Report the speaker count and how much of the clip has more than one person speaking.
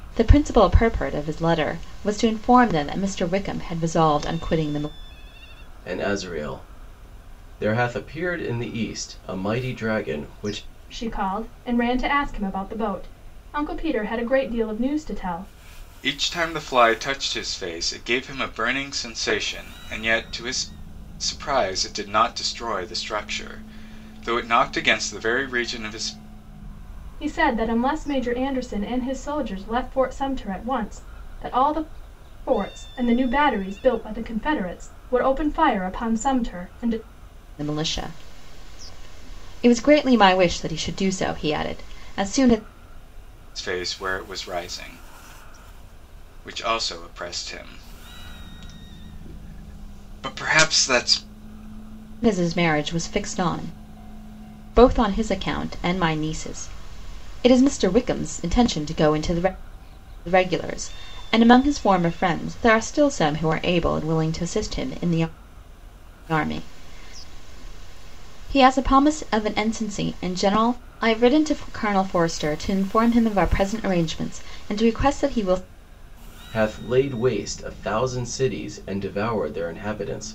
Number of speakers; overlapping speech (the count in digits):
4, no overlap